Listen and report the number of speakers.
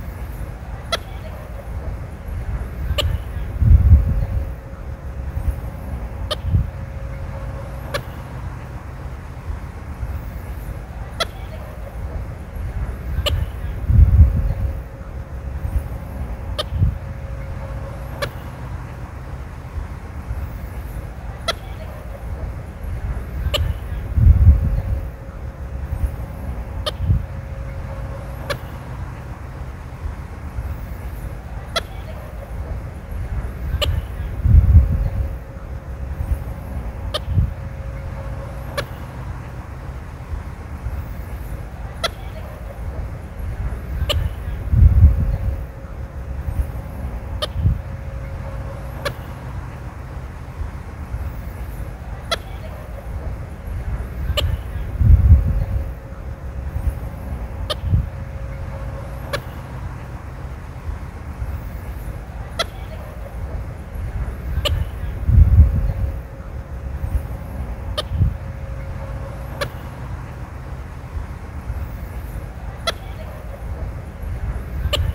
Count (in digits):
0